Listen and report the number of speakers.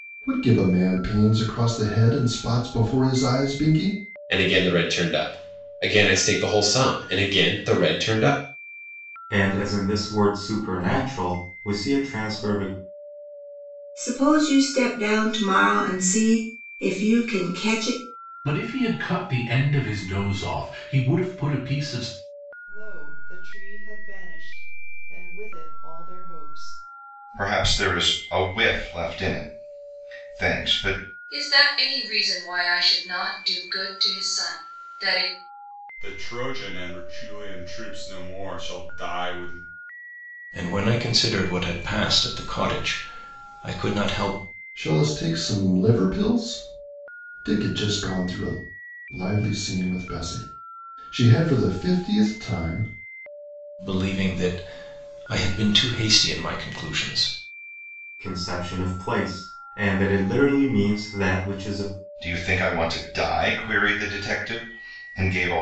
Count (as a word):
ten